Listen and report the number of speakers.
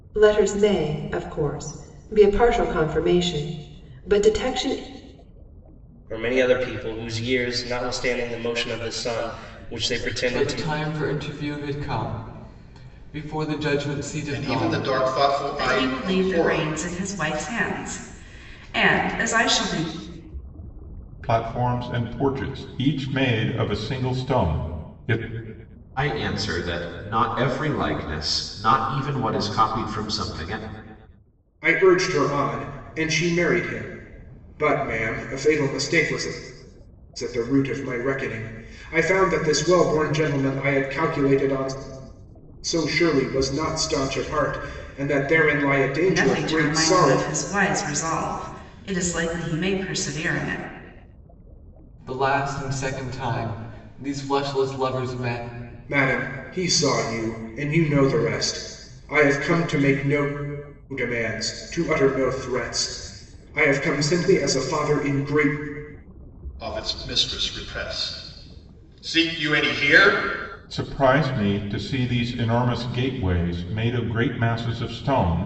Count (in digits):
8